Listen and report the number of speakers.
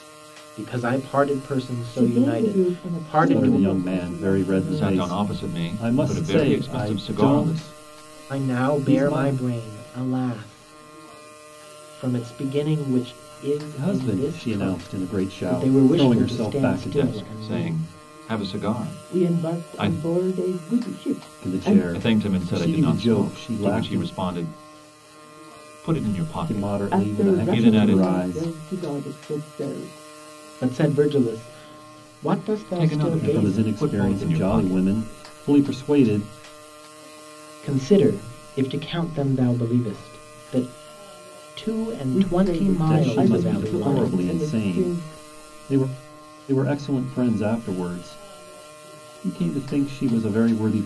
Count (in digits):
4